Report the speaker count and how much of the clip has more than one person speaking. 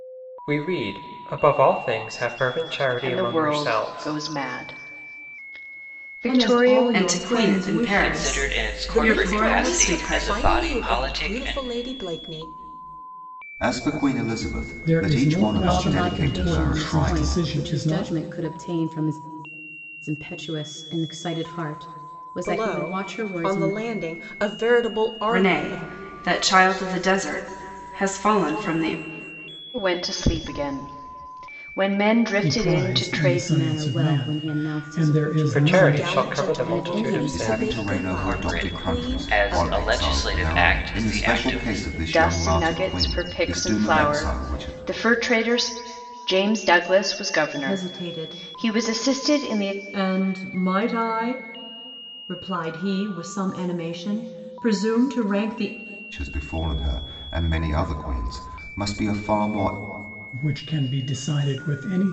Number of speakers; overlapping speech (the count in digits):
9, about 43%